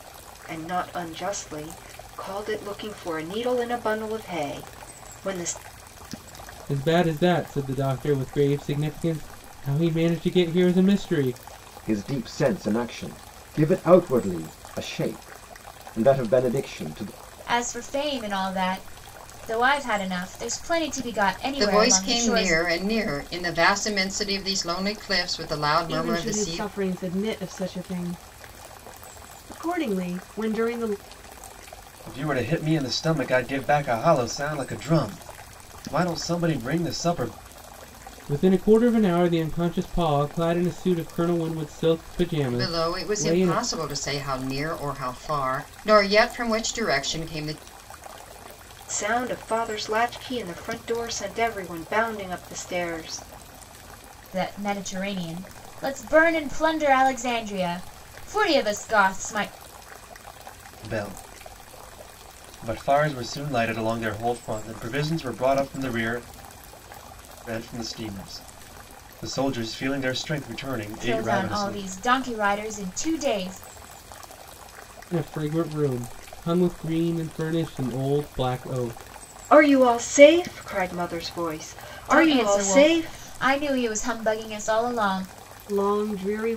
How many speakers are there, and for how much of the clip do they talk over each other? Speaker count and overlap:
seven, about 6%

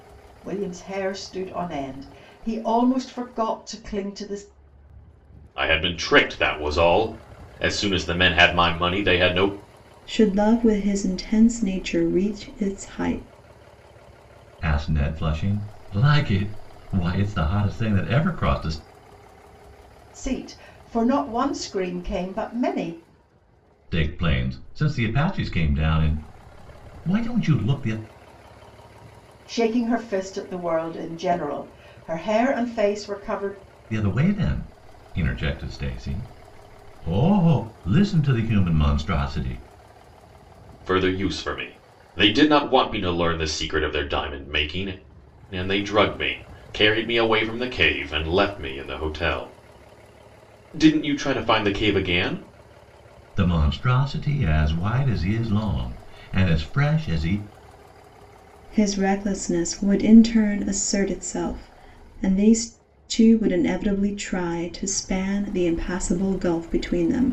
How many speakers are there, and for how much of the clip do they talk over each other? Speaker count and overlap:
four, no overlap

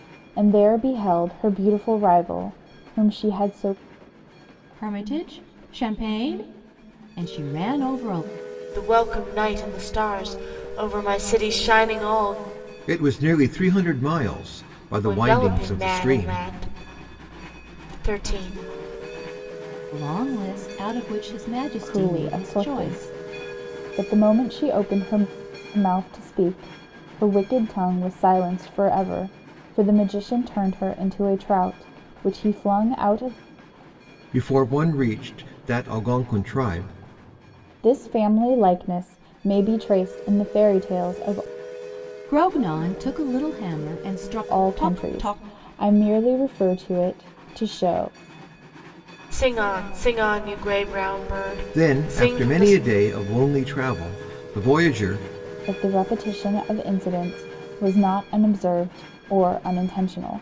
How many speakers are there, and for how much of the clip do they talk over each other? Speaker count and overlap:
four, about 8%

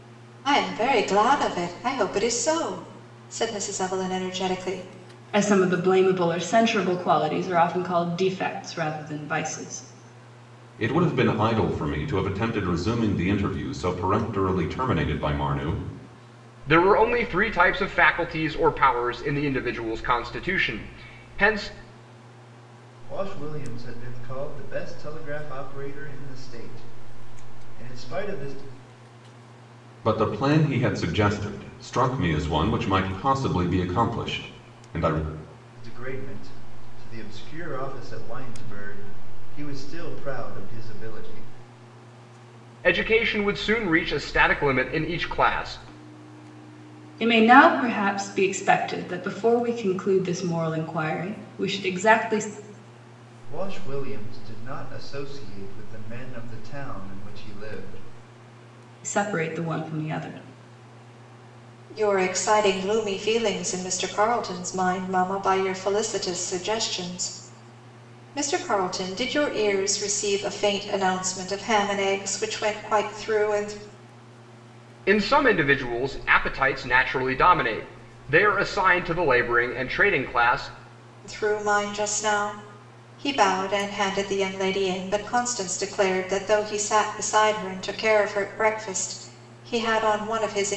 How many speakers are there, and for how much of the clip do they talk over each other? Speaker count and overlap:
five, no overlap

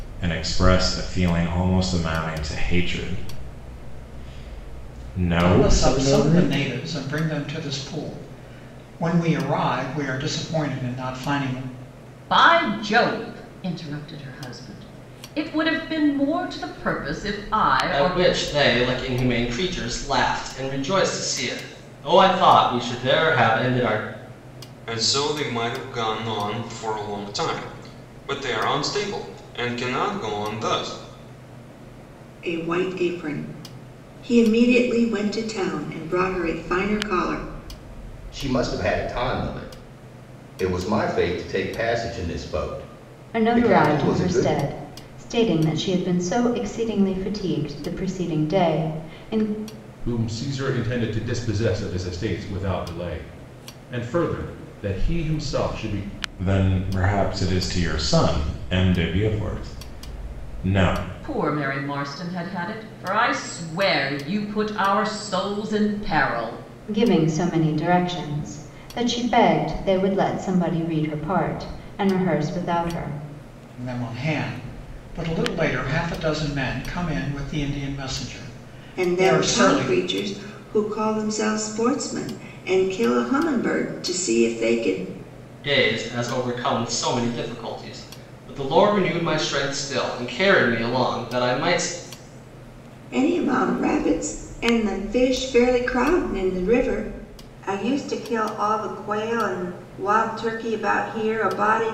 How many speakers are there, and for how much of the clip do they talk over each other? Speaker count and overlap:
nine, about 4%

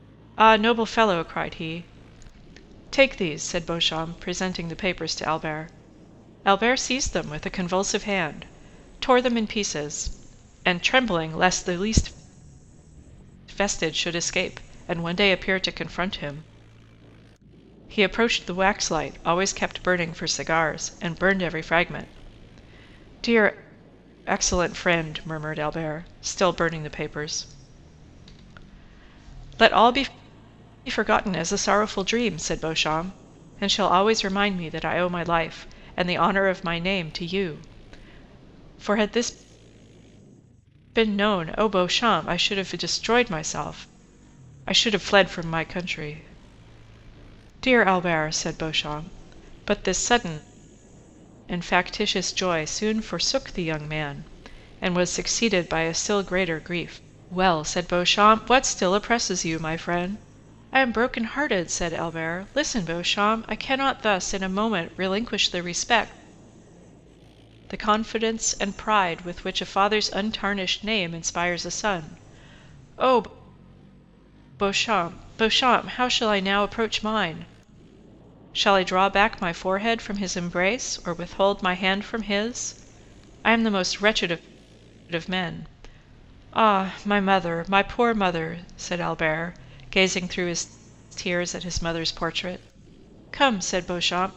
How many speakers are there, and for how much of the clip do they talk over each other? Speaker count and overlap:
one, no overlap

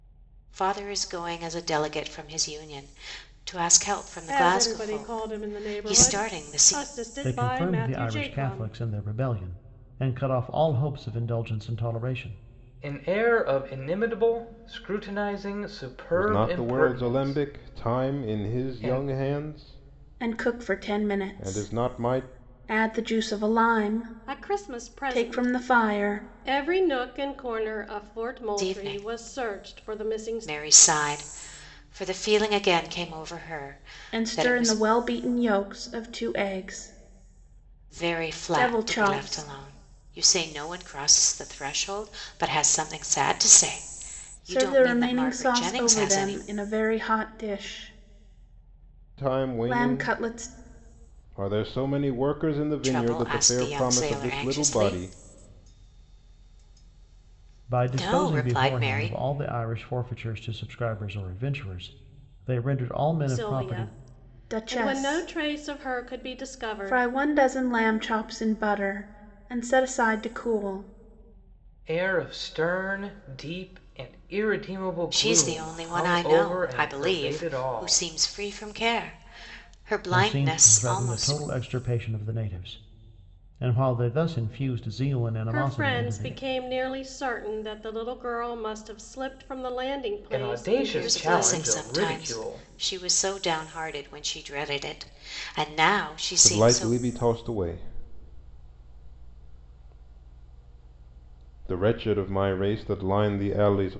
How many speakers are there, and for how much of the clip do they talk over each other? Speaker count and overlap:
six, about 33%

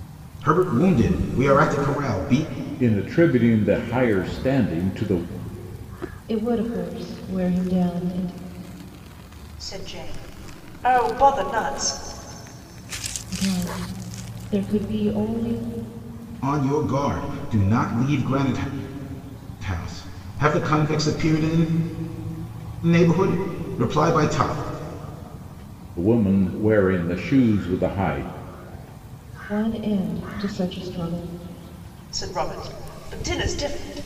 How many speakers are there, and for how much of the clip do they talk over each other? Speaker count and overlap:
four, no overlap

